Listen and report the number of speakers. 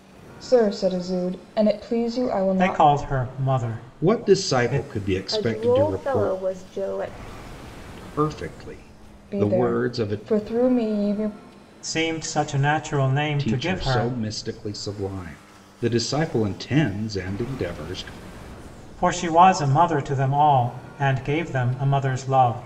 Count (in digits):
4